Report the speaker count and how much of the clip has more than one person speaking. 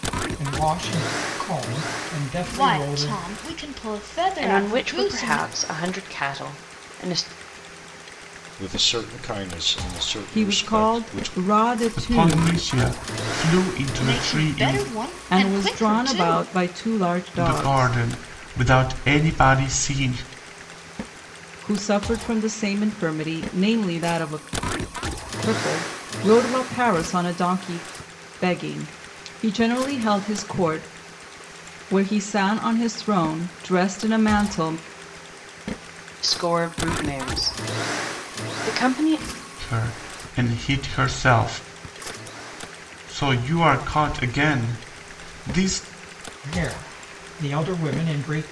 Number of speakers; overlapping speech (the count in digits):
6, about 13%